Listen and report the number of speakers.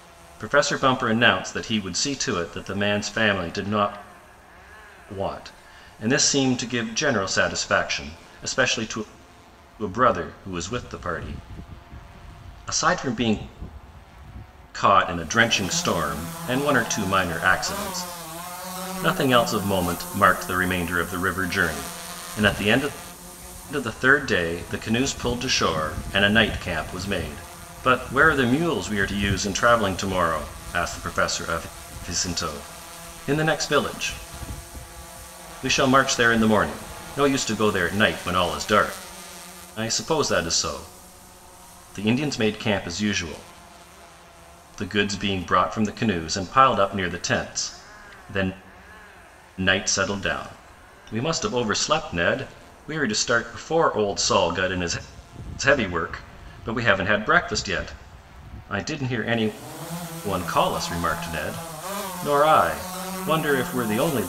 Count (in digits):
1